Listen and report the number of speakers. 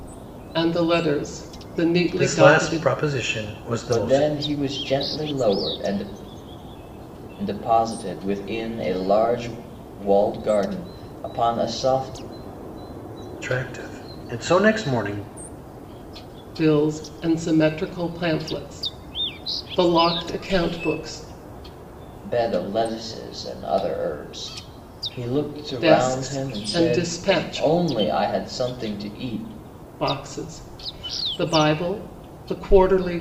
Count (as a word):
three